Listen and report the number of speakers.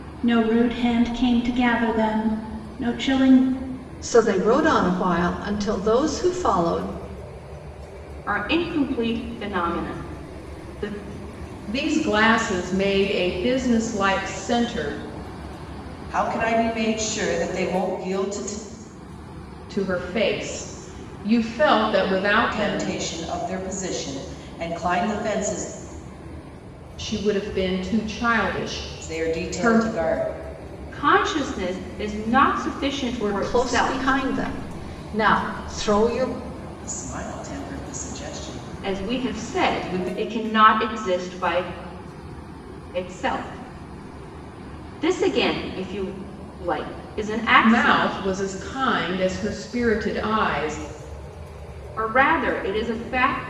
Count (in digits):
5